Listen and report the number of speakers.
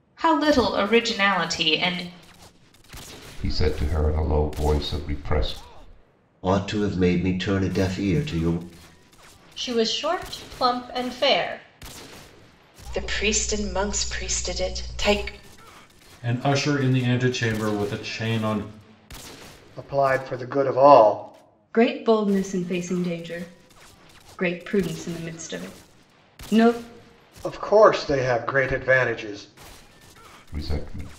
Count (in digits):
8